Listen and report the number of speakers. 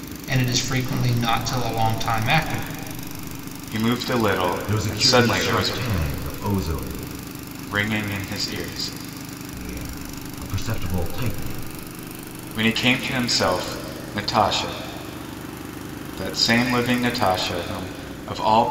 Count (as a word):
three